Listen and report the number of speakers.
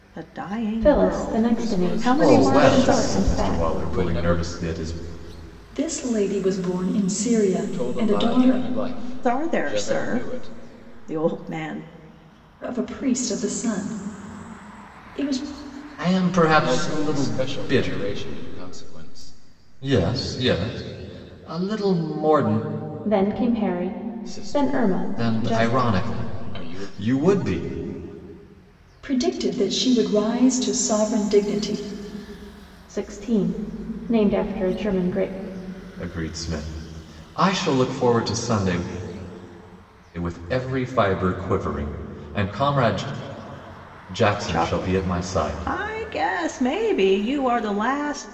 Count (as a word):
five